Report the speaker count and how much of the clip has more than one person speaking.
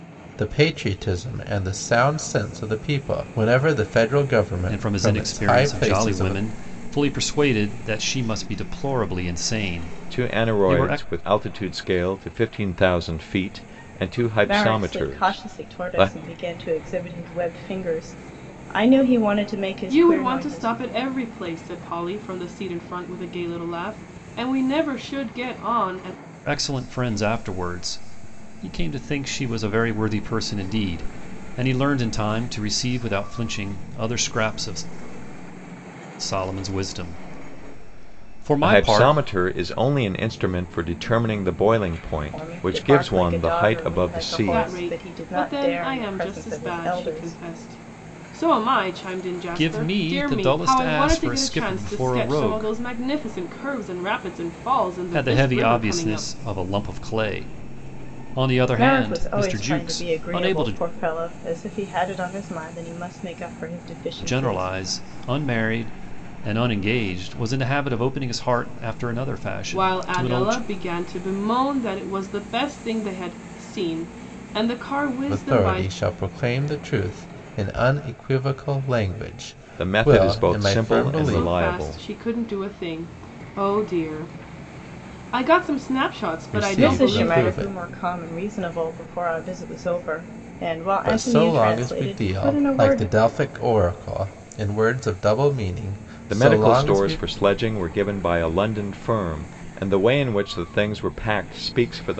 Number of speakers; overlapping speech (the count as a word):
five, about 26%